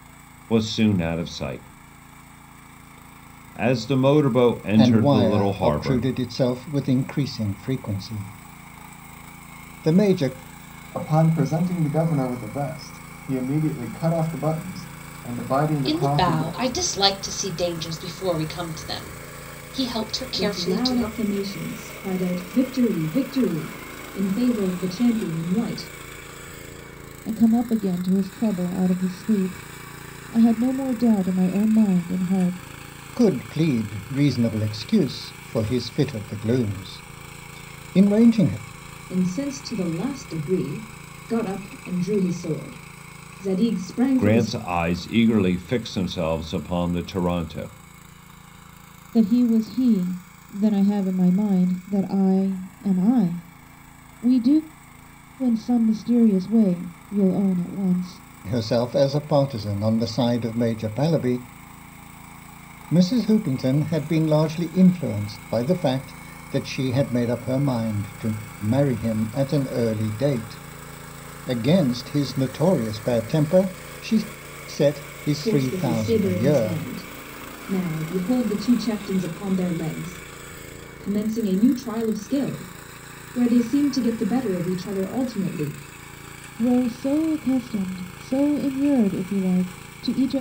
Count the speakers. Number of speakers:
six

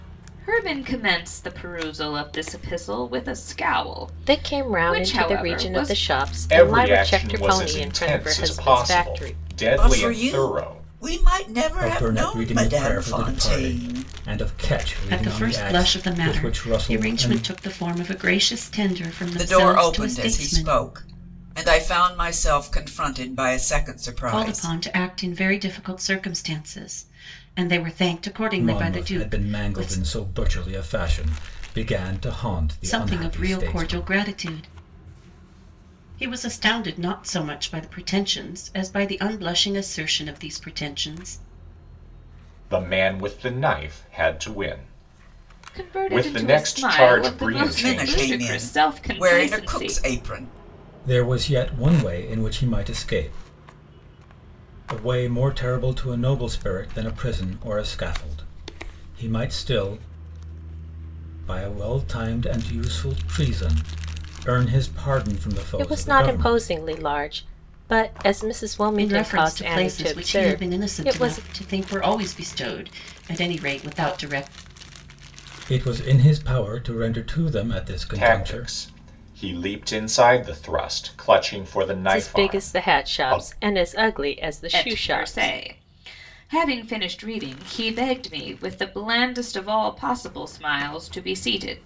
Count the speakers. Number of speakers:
six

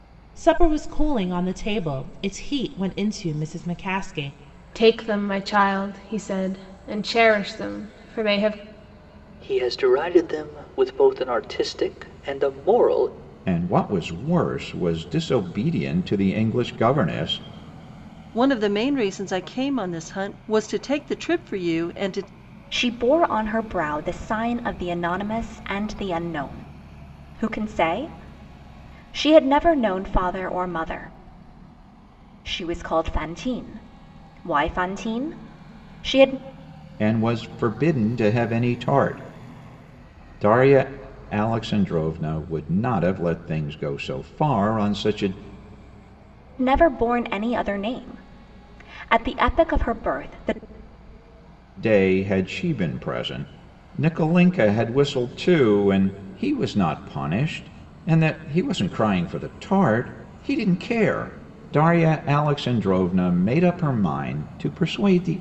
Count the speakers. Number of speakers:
six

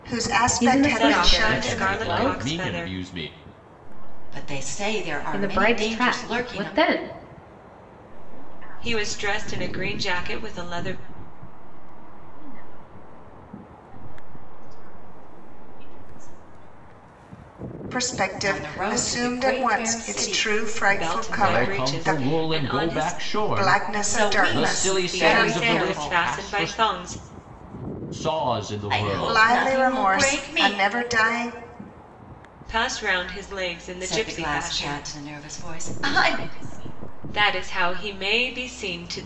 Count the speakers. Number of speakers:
six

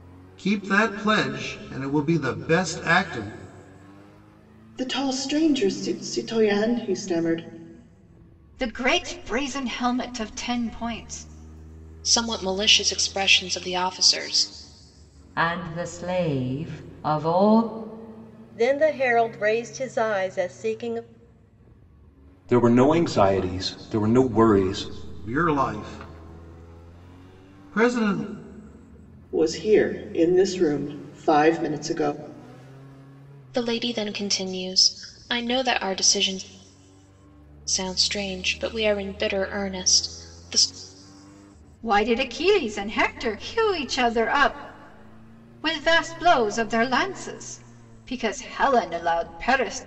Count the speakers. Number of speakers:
seven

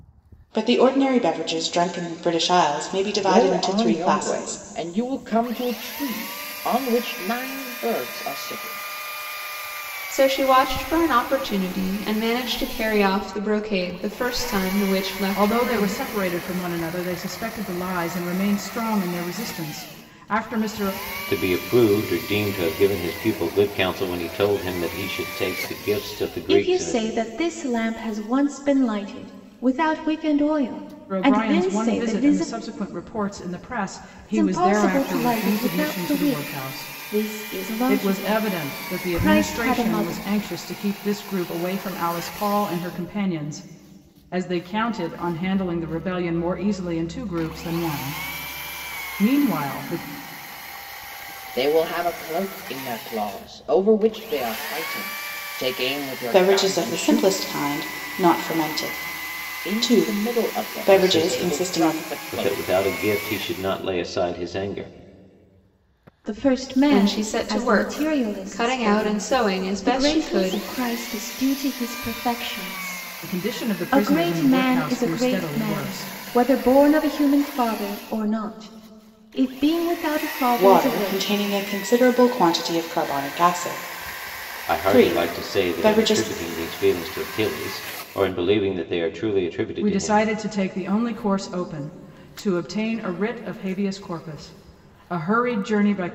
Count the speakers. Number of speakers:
six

